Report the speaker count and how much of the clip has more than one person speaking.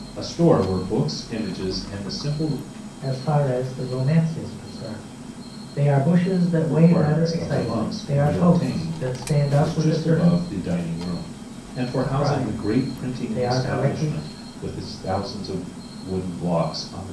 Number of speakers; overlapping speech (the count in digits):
2, about 31%